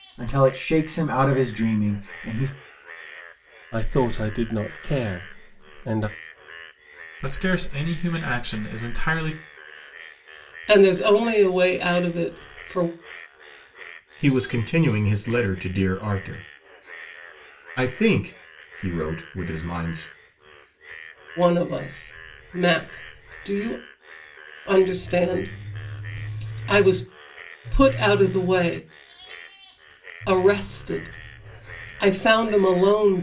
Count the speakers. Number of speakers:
five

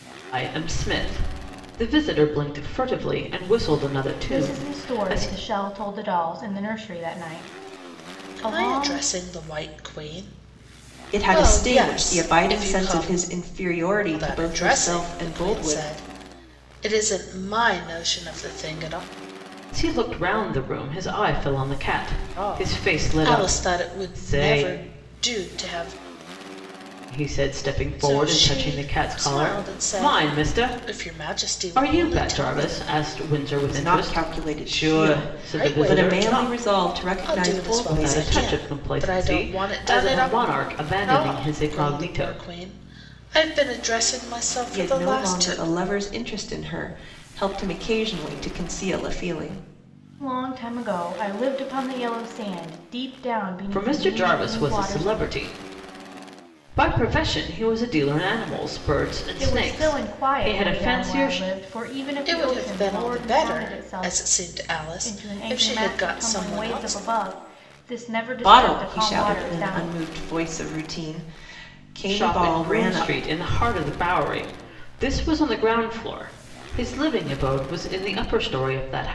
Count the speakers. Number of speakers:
four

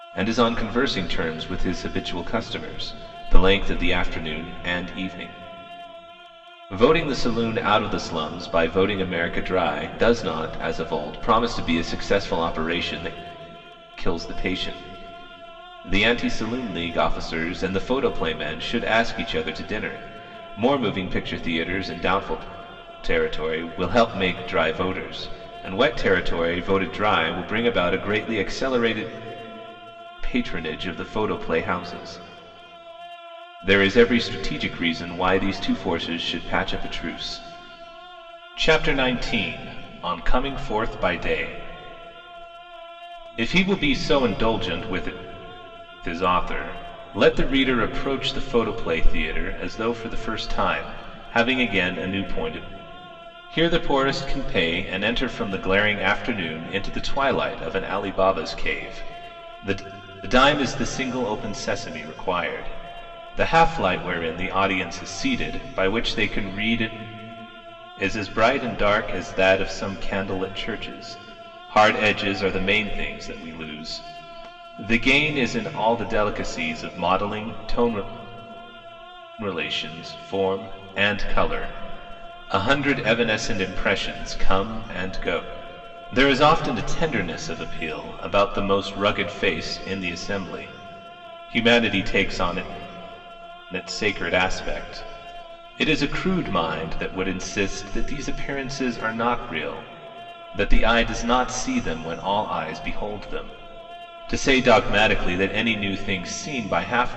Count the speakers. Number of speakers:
one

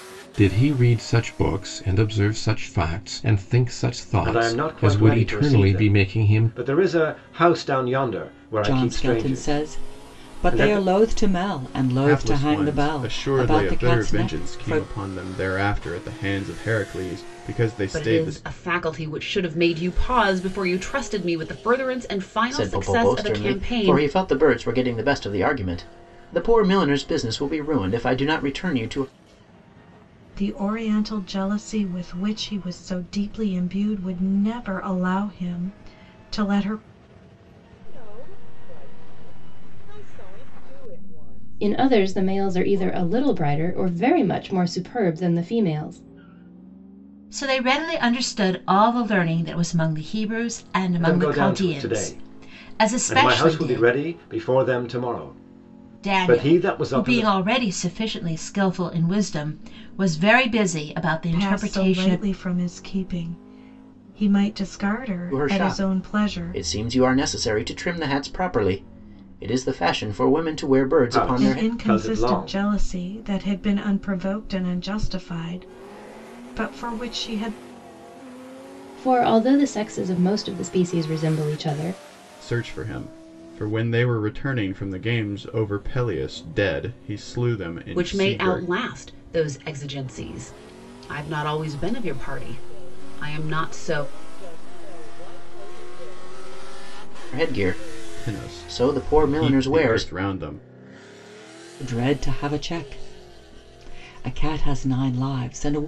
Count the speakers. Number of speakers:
ten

